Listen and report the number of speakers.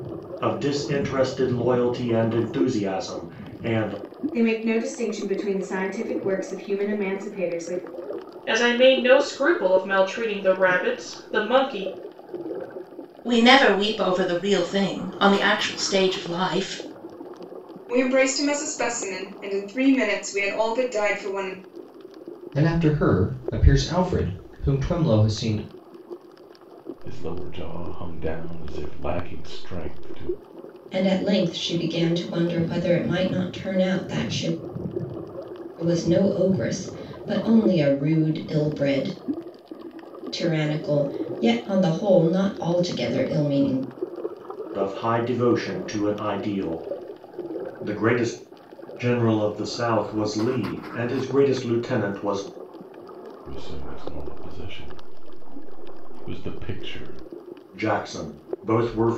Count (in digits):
8